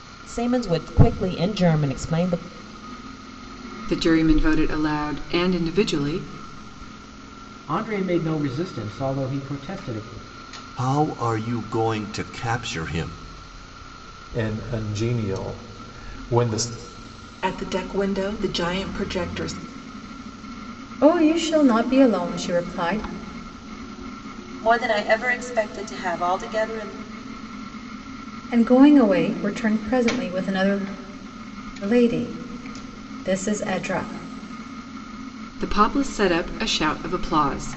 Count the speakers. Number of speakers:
8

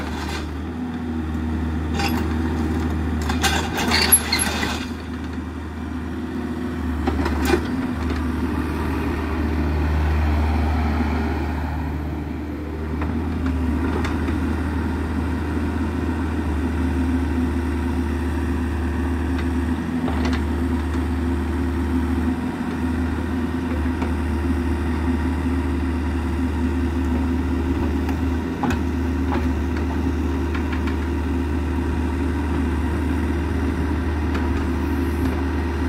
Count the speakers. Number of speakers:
0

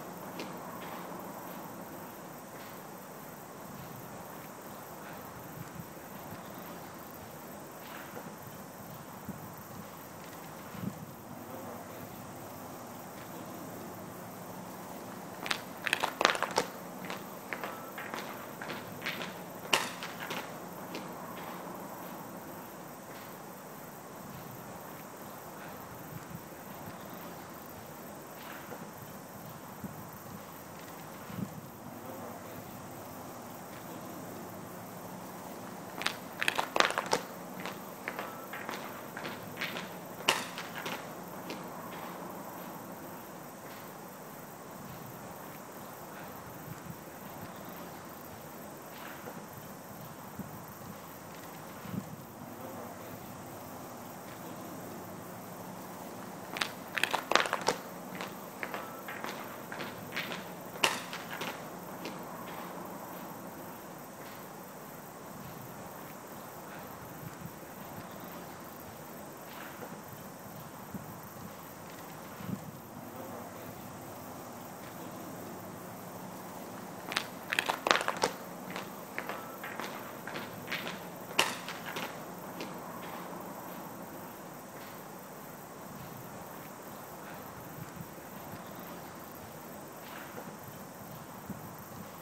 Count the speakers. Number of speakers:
0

